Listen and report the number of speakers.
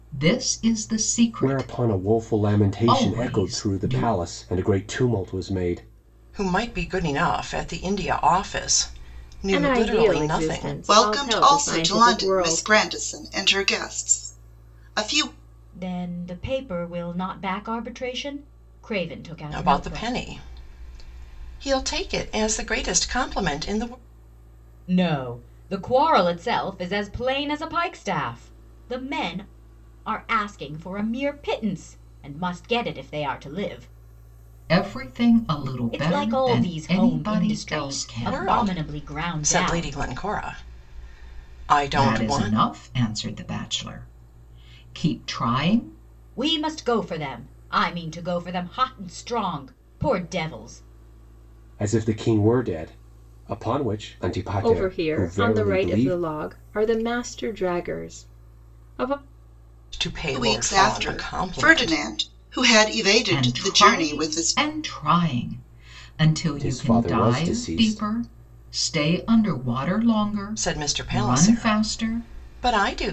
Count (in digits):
6